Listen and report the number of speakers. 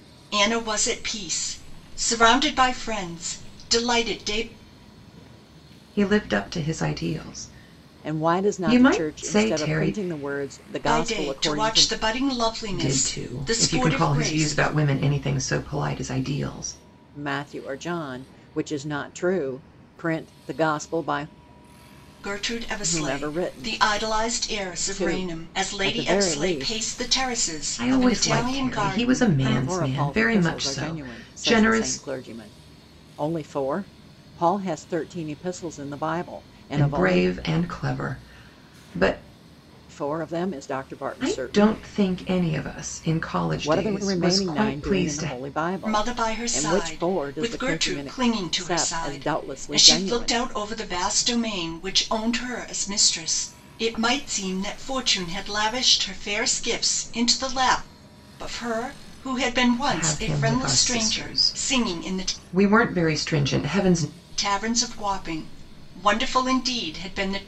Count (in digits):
3